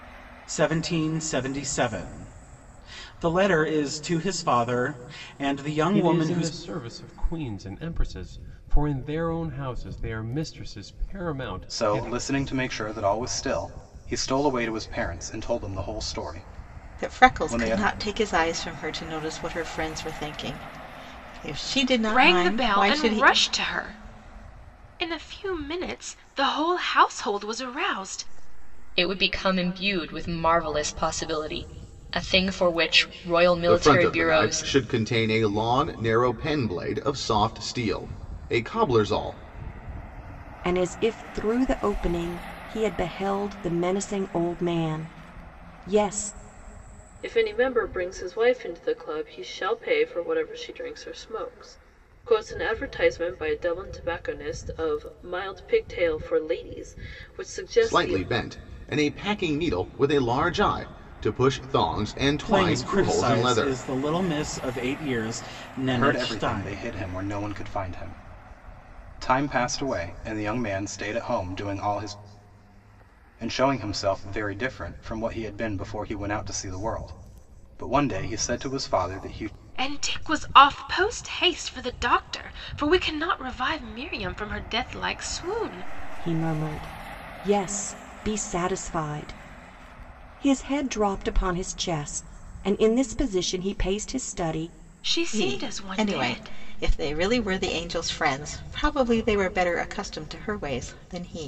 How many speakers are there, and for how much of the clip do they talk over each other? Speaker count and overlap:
9, about 8%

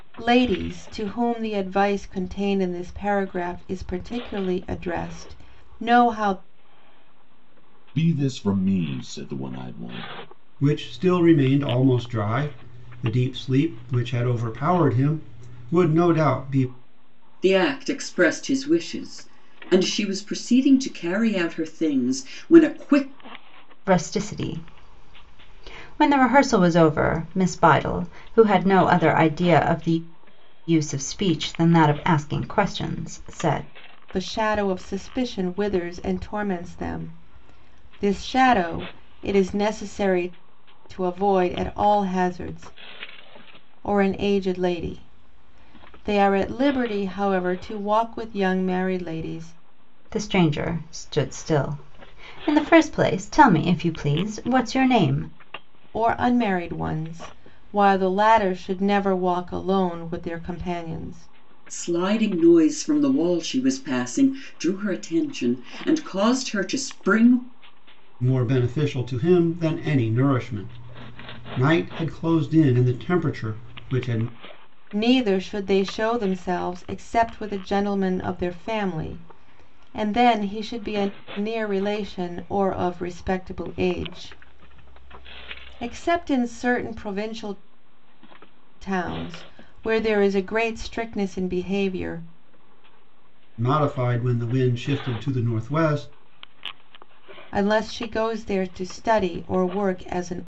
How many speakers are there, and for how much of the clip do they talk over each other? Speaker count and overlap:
5, no overlap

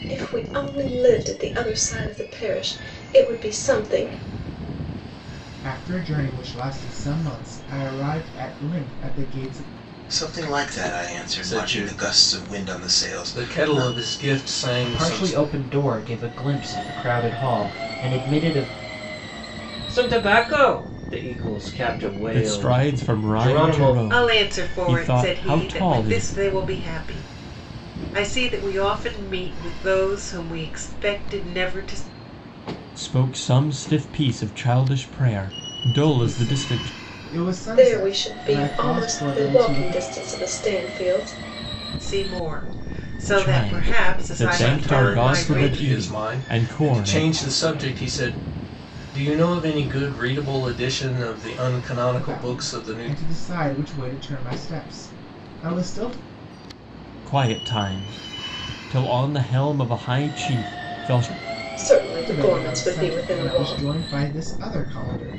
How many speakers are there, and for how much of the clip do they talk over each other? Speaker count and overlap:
8, about 26%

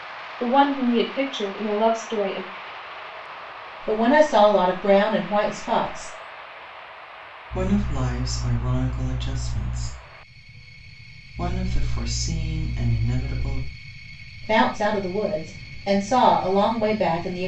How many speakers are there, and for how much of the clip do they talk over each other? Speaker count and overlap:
3, no overlap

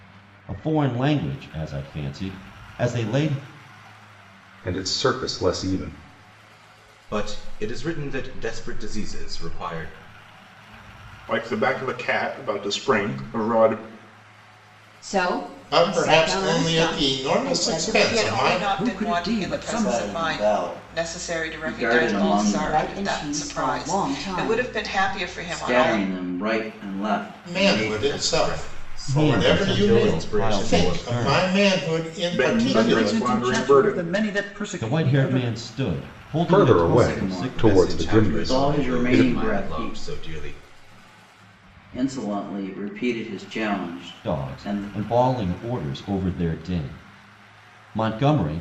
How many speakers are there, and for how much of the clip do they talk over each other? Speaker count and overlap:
9, about 41%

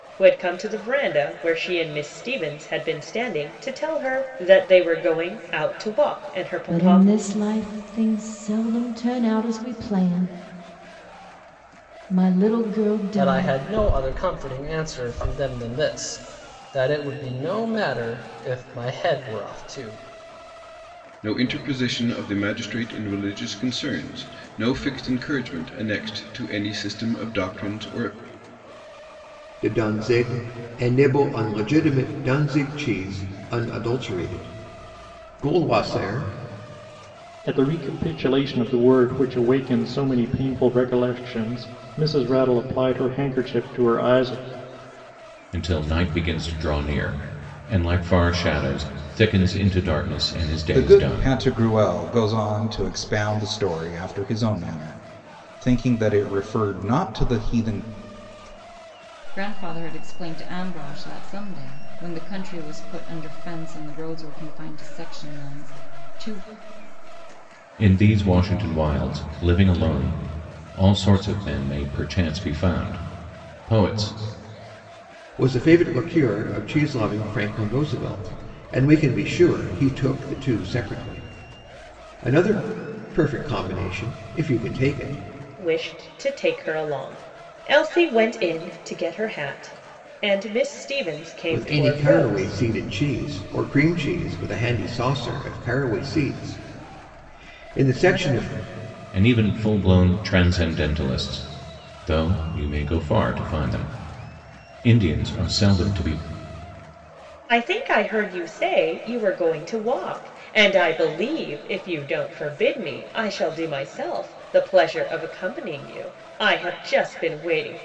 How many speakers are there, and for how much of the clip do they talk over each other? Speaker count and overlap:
9, about 2%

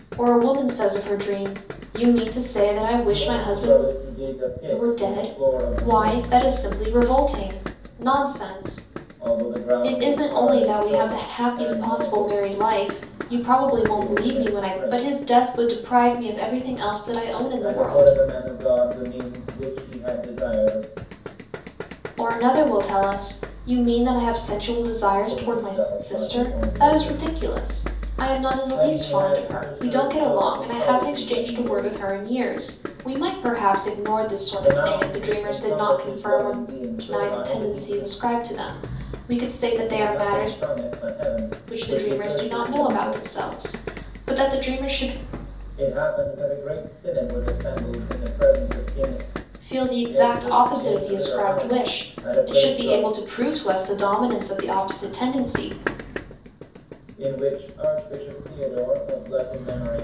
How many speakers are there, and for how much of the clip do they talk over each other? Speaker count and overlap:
2, about 36%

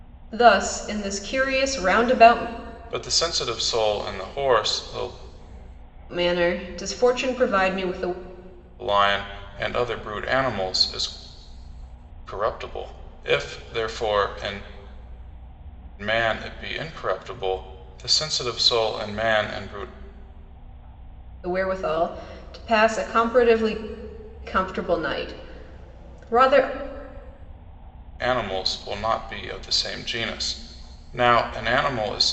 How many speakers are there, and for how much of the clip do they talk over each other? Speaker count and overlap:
2, no overlap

